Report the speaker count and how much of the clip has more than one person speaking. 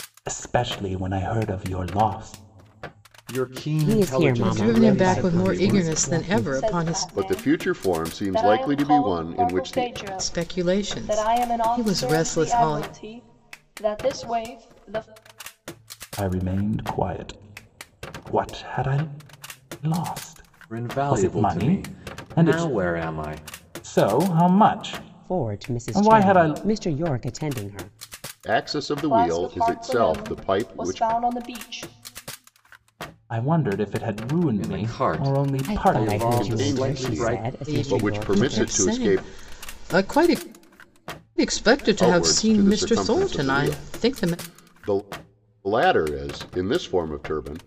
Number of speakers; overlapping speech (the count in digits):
6, about 45%